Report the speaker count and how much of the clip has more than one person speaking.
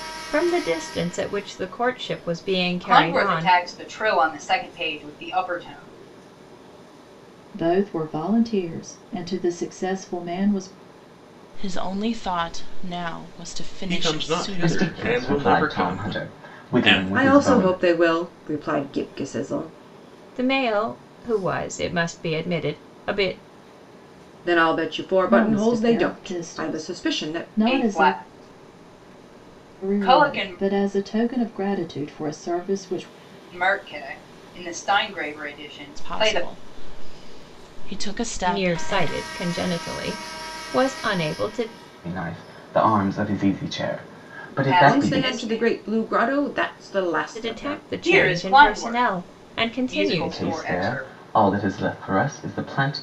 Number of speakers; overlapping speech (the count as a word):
seven, about 28%